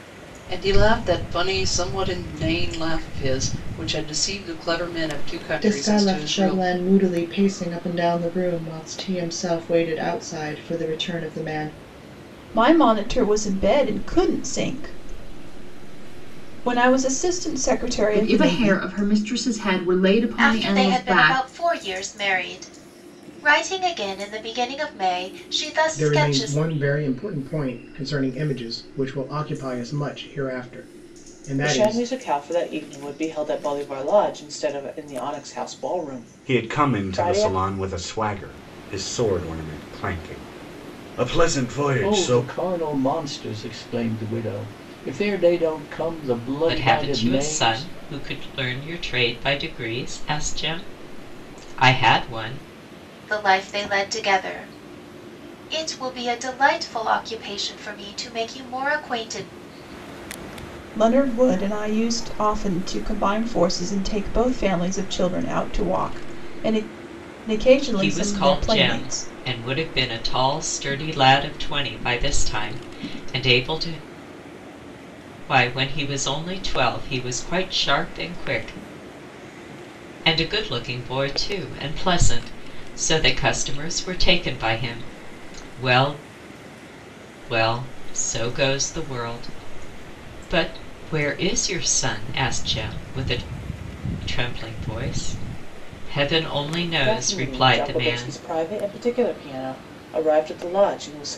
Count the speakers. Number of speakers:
ten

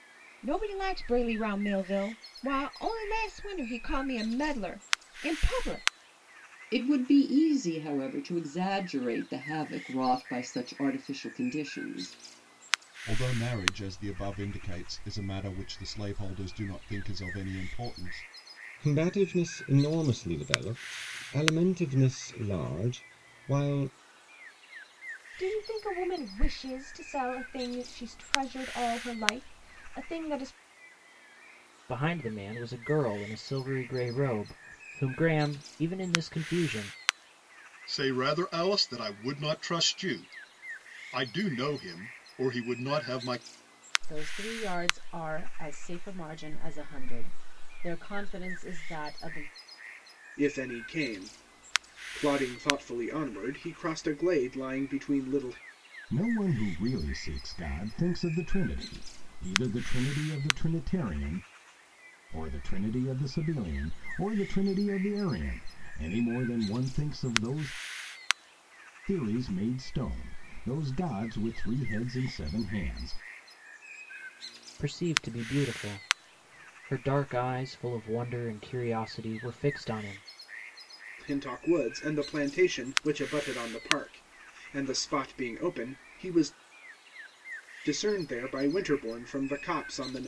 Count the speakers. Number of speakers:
ten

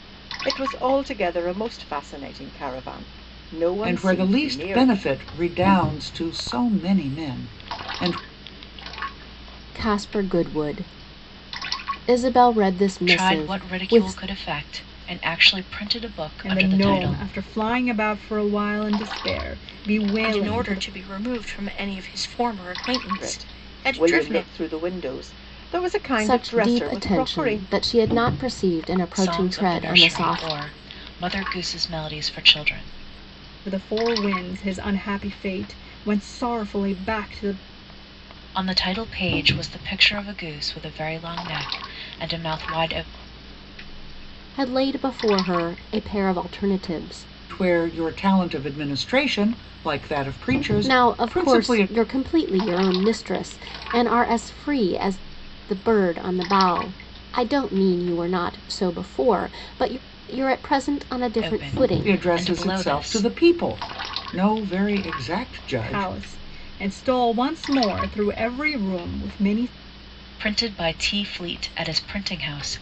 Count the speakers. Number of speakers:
six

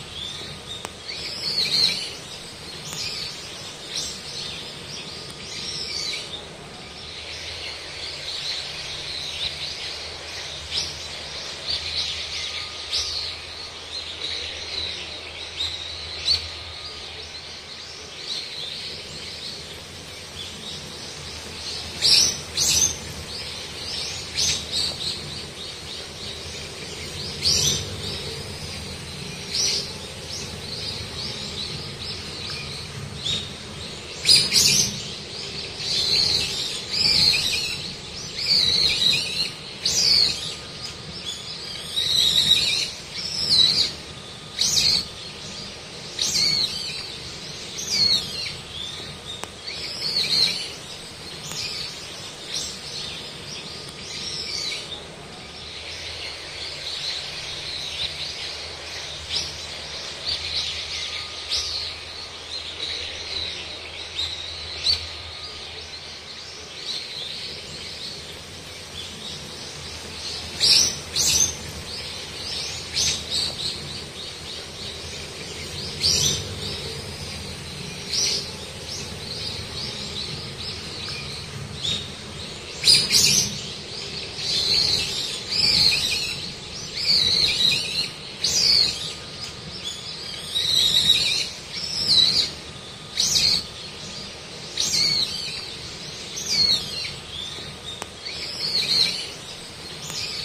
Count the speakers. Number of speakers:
zero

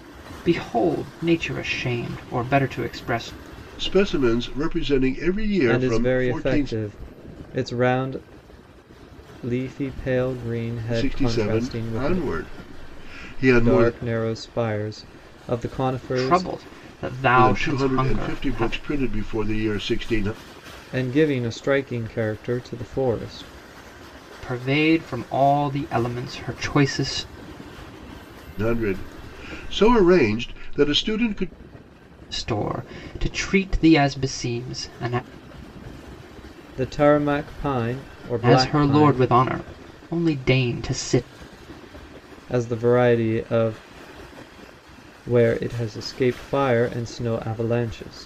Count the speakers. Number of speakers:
three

